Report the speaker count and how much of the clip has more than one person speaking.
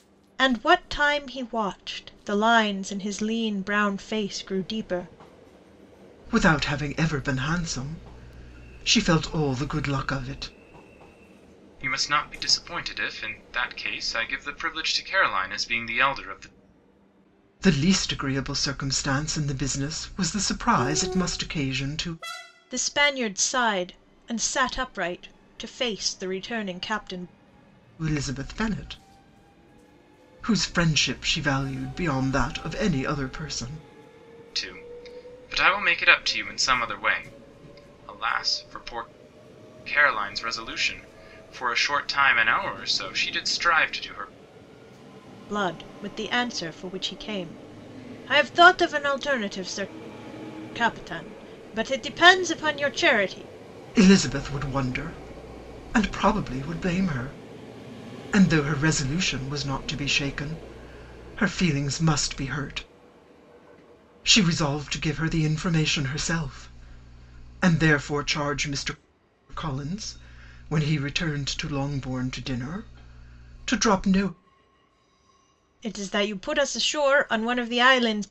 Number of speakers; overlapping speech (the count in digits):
3, no overlap